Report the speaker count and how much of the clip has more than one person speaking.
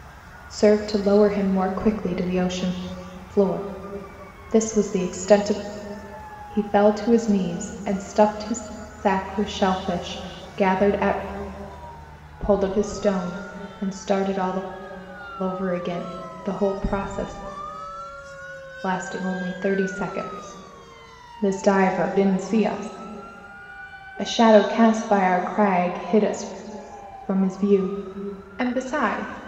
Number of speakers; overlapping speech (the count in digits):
1, no overlap